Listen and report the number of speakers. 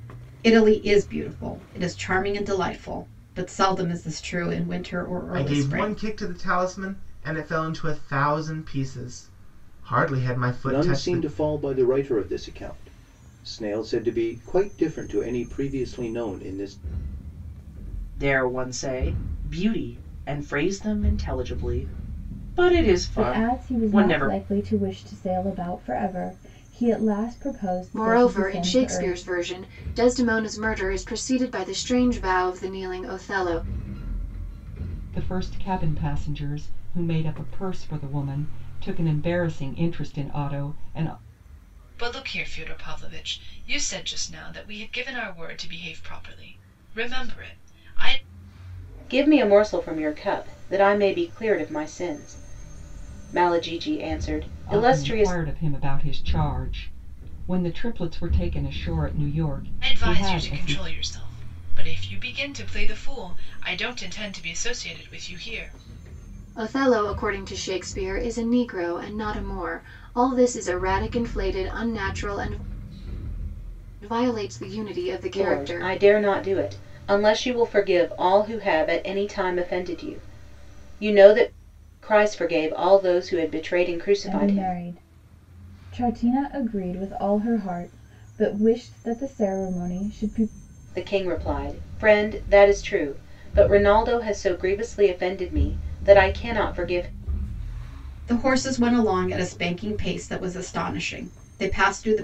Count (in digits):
9